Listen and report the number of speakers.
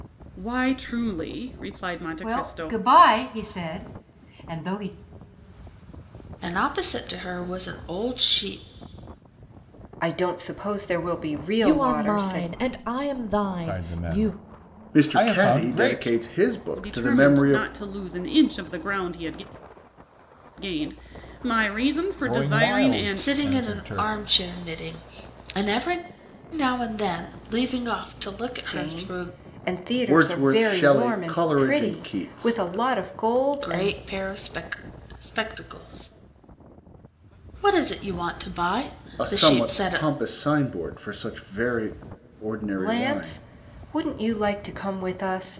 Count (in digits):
7